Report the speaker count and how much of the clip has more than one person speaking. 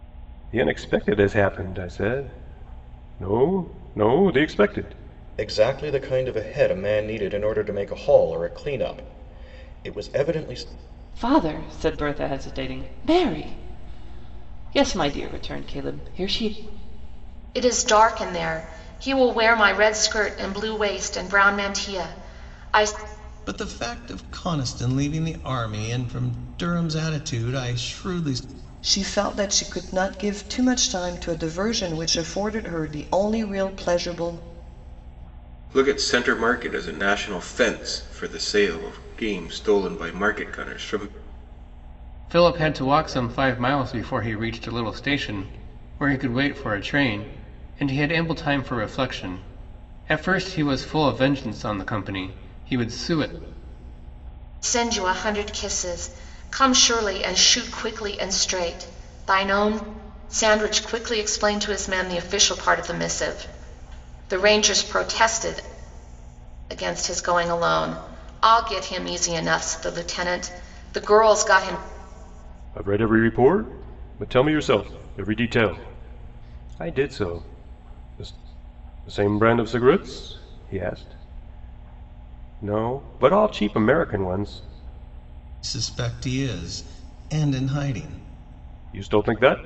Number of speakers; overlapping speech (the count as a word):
eight, no overlap